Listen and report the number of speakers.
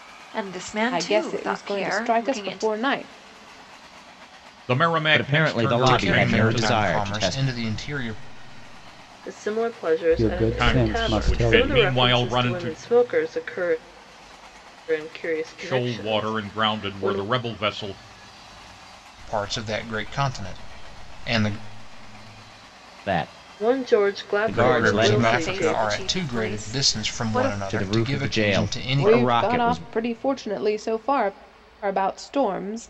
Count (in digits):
7